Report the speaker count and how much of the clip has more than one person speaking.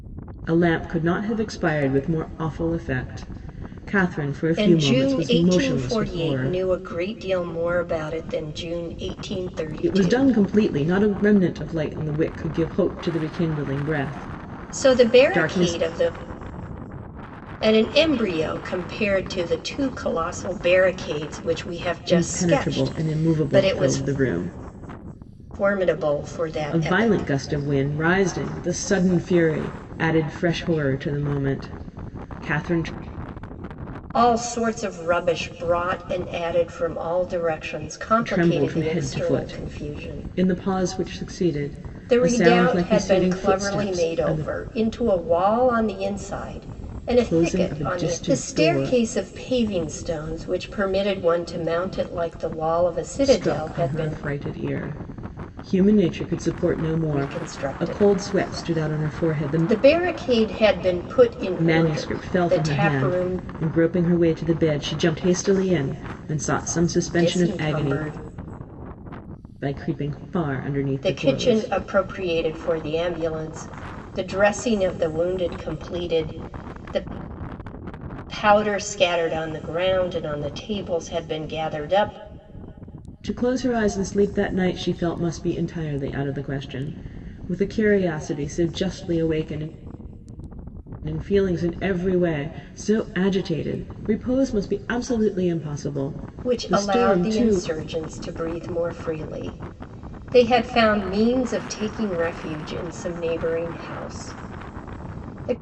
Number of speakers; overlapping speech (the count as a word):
two, about 21%